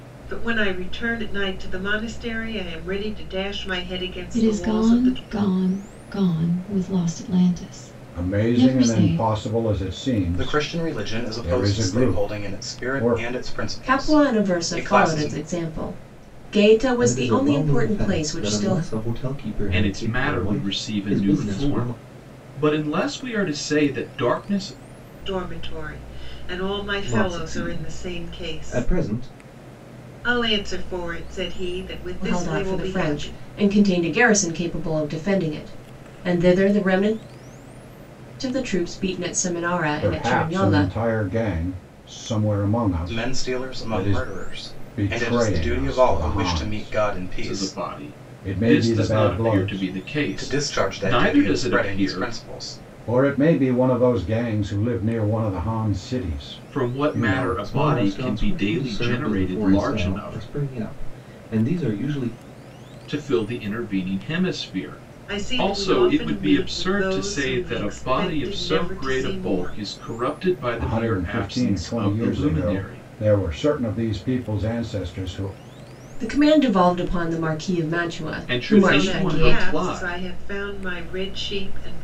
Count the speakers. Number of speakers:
seven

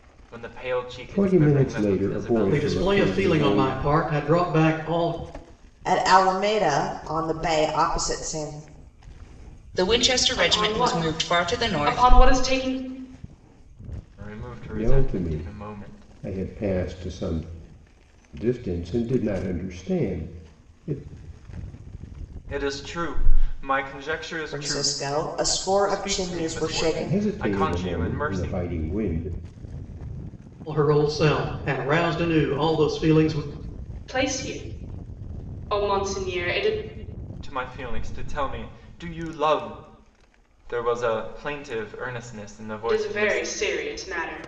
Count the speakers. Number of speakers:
six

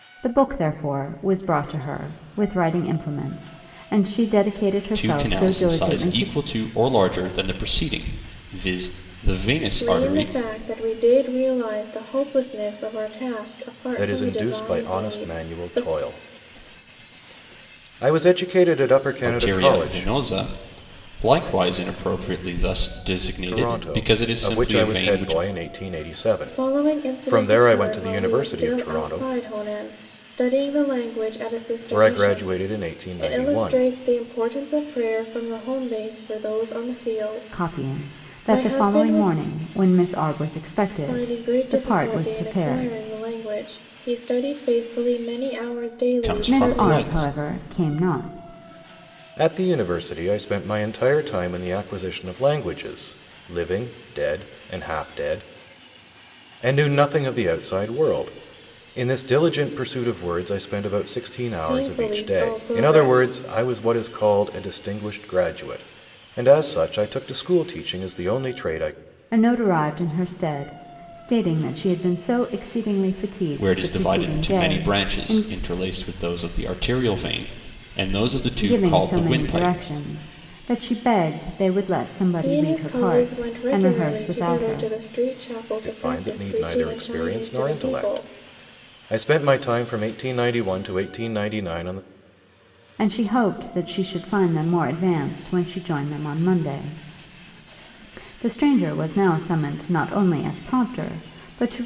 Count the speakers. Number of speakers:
four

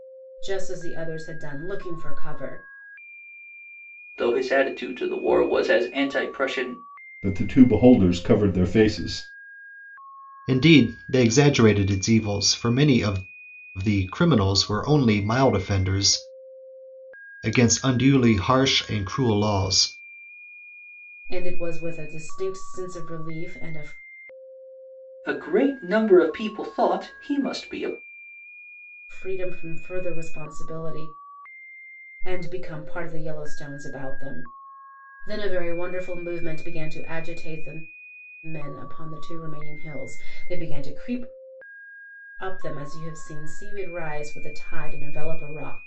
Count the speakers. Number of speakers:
four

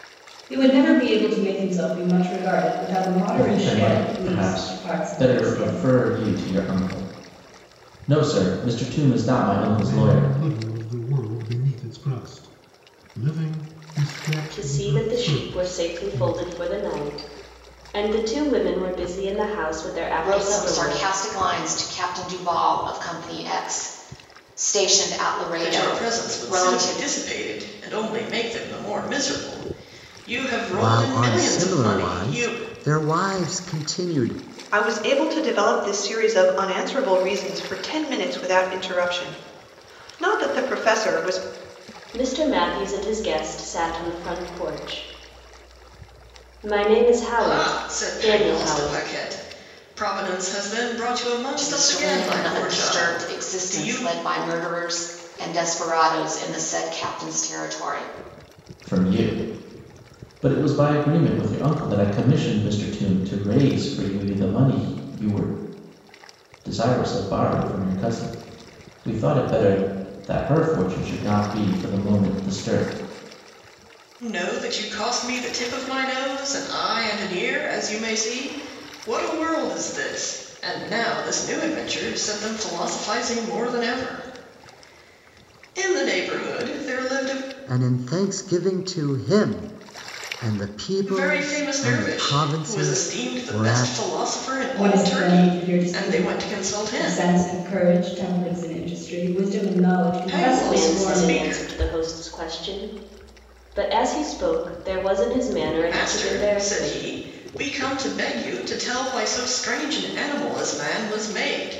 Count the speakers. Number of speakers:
eight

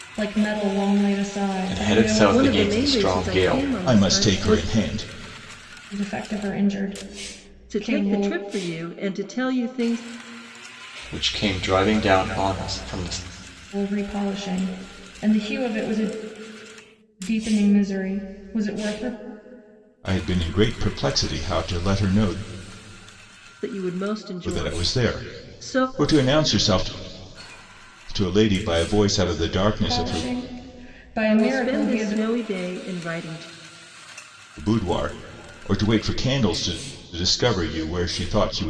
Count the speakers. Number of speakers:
four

